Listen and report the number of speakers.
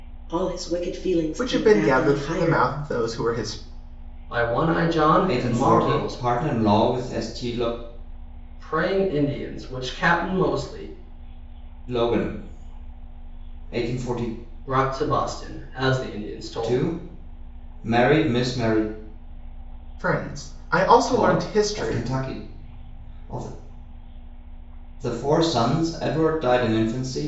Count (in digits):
4